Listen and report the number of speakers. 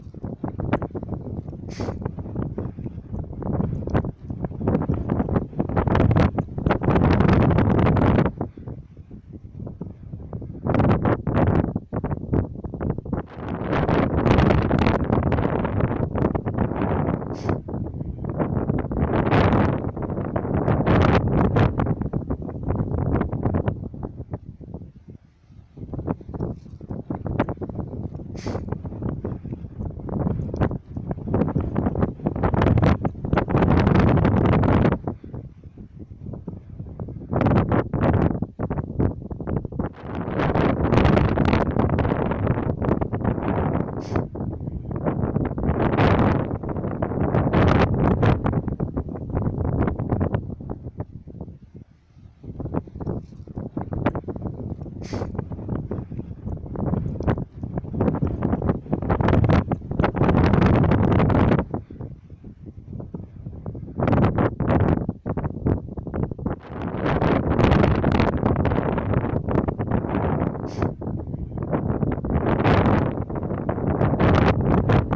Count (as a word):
zero